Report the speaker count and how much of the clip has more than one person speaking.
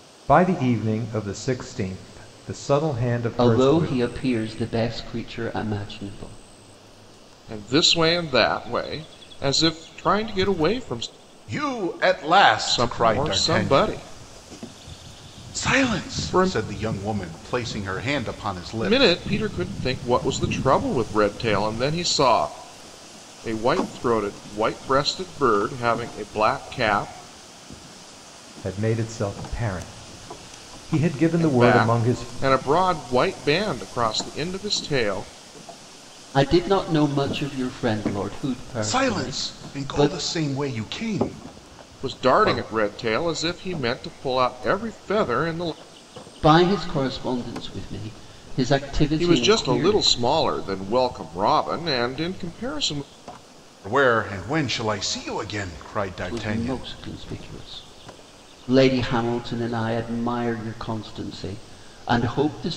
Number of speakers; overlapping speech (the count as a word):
four, about 13%